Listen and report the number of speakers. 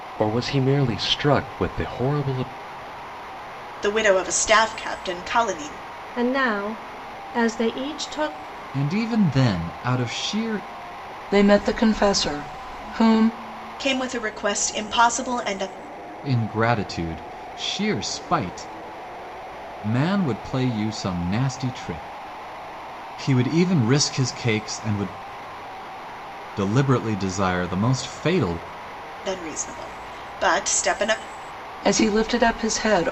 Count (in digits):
5